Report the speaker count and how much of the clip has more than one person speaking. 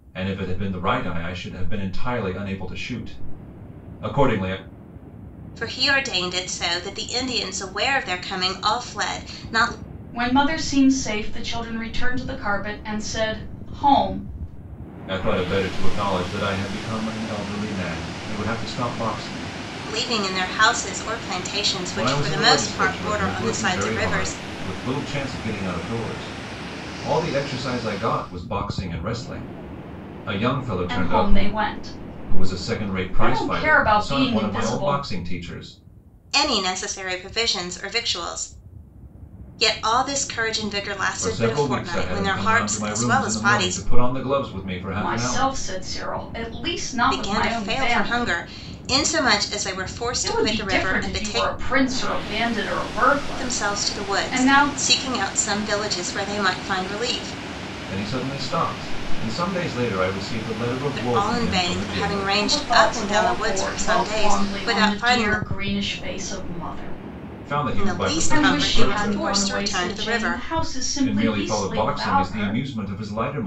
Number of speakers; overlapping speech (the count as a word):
three, about 30%